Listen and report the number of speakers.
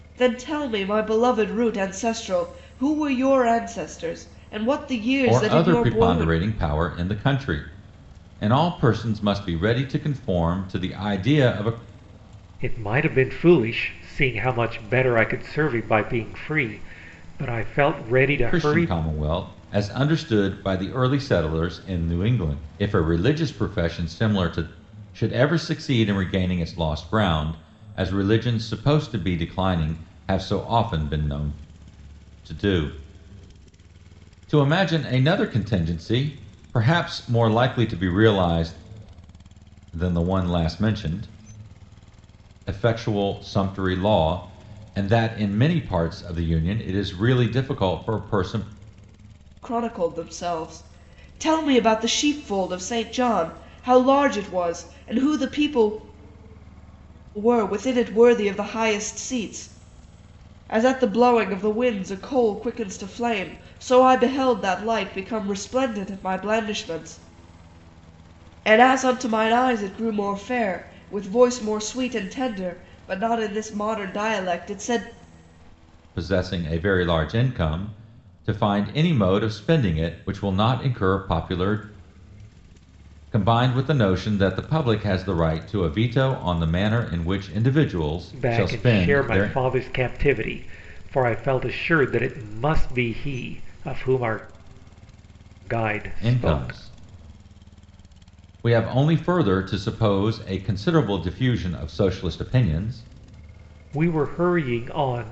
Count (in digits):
3